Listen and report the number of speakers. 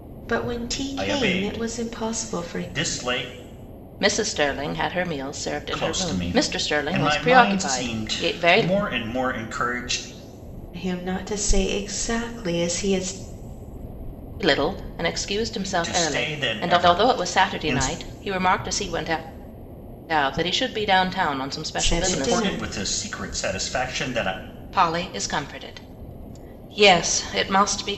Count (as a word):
three